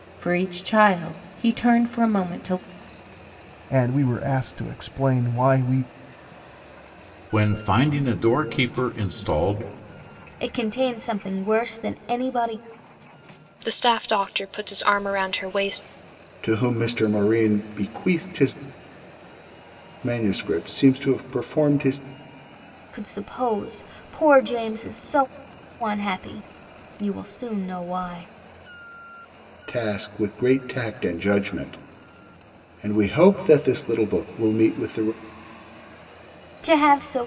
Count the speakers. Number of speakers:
6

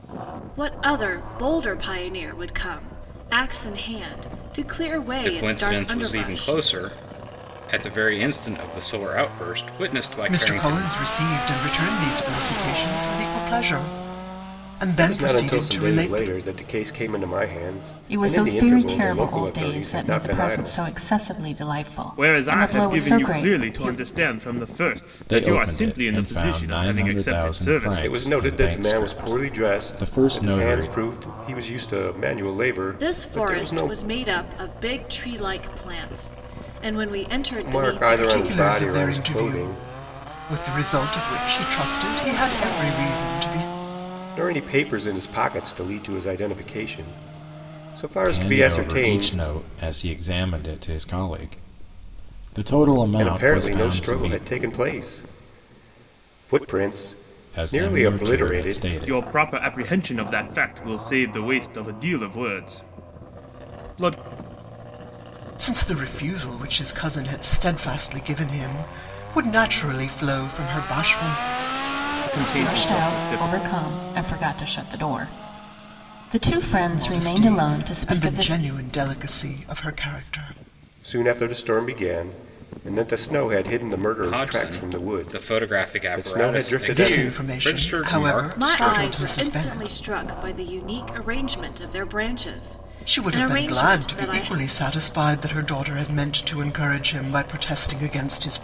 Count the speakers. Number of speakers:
7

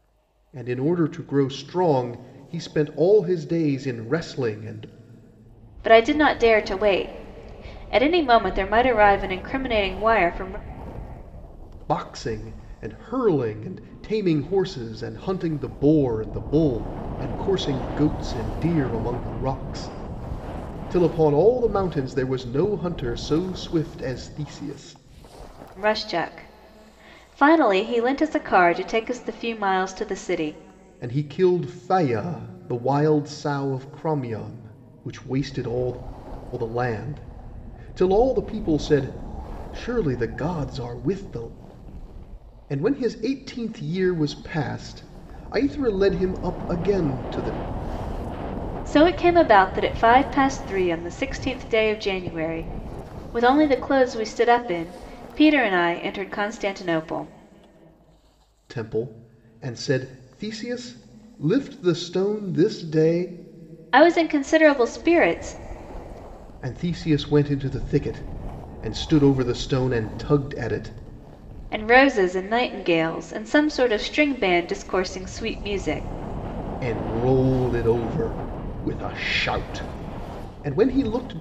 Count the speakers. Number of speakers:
2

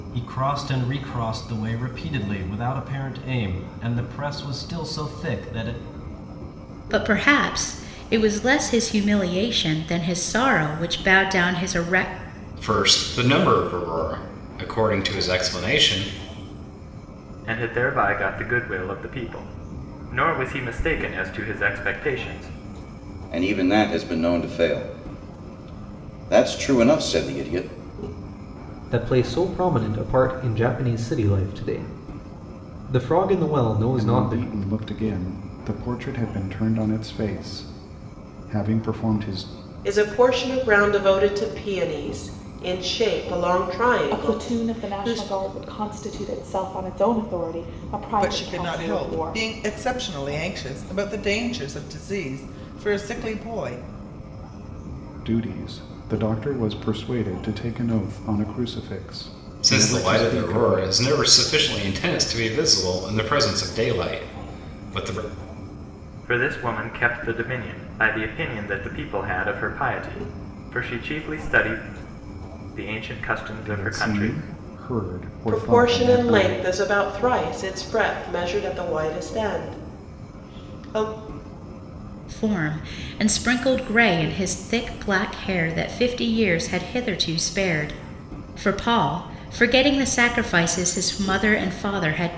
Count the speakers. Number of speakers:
10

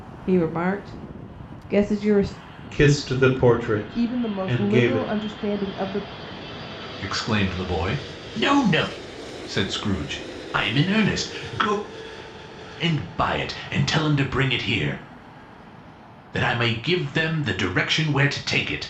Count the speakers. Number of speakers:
4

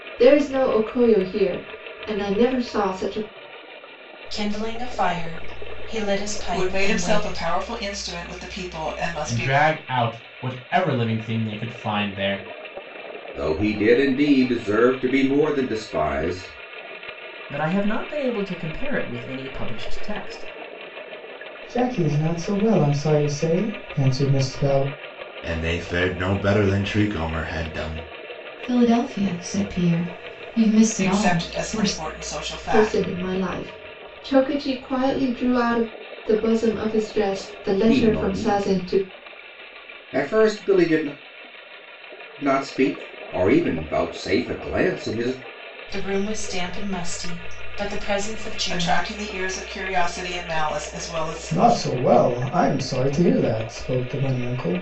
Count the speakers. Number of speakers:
9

